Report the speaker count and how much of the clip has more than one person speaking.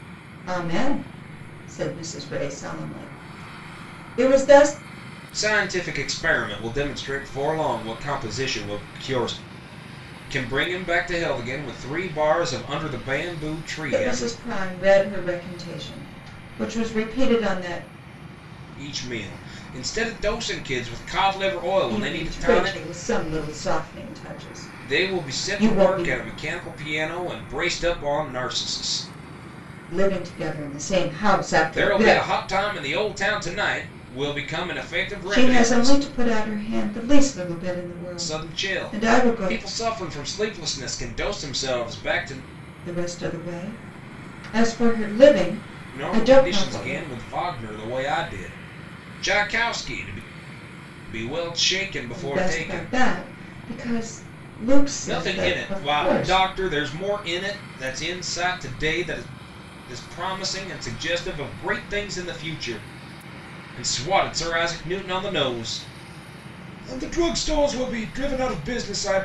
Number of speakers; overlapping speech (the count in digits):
2, about 13%